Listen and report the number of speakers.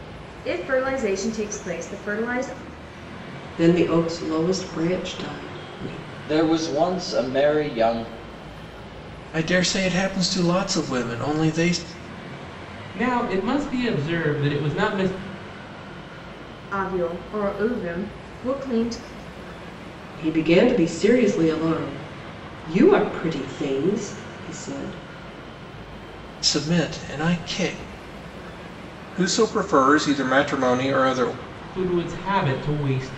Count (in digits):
5